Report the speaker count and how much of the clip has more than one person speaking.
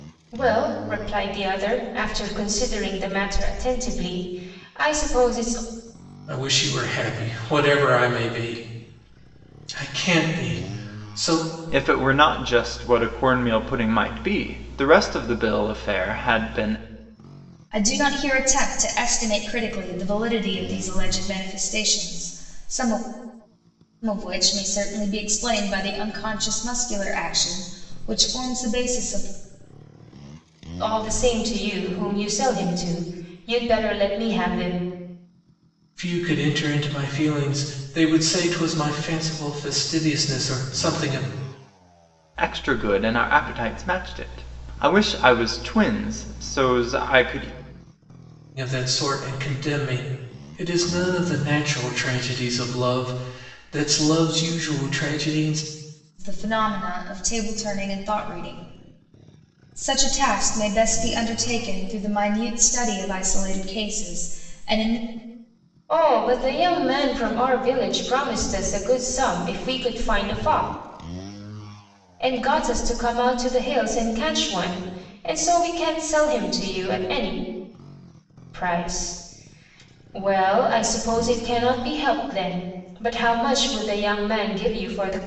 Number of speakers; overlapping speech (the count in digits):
4, no overlap